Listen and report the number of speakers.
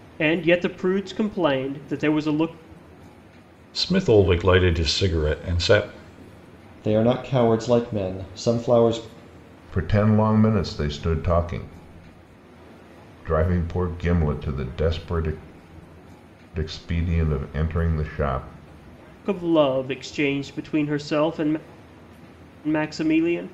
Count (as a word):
four